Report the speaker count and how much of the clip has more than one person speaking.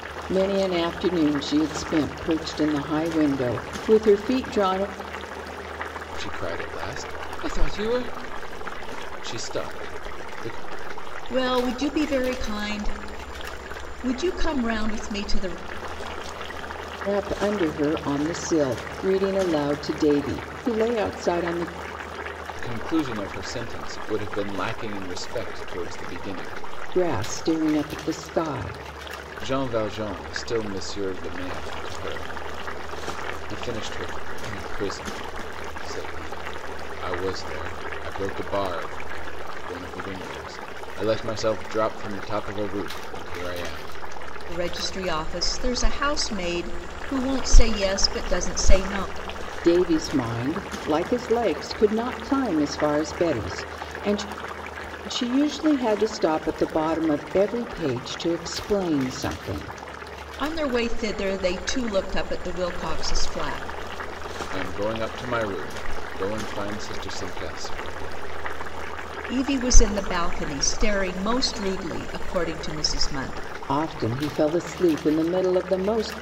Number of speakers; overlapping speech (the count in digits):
3, no overlap